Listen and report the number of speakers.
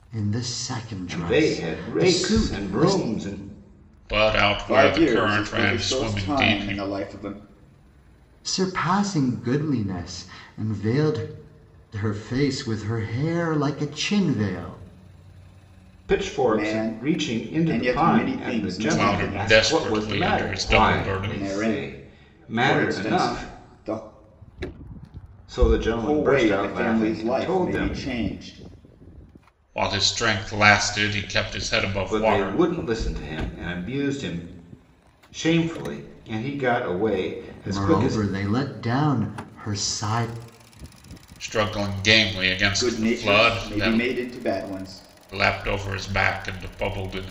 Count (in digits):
4